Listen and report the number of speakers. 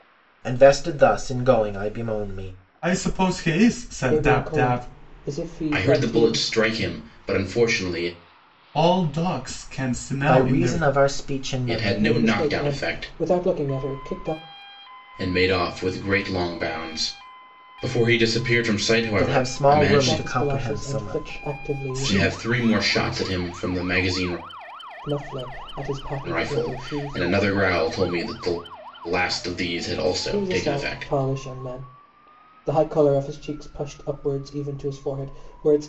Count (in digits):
4